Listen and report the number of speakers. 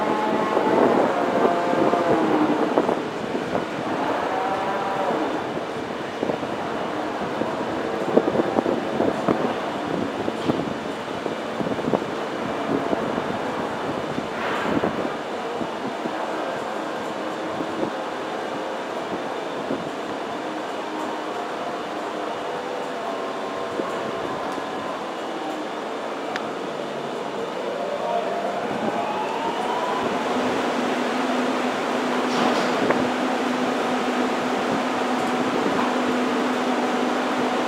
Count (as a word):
zero